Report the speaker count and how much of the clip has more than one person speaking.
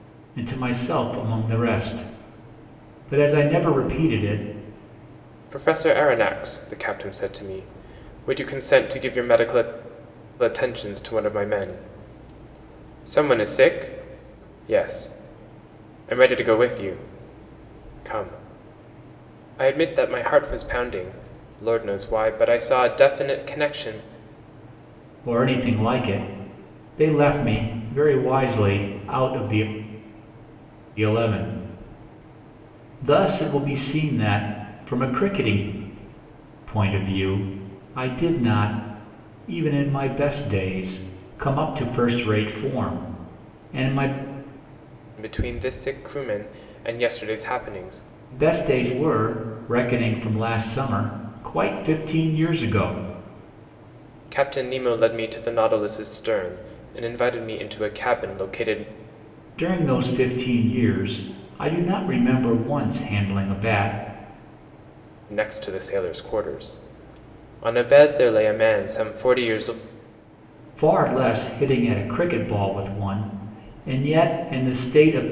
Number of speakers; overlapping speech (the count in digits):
2, no overlap